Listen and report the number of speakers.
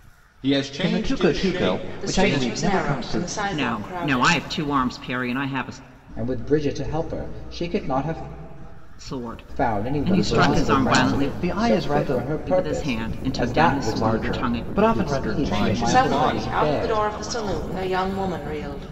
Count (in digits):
5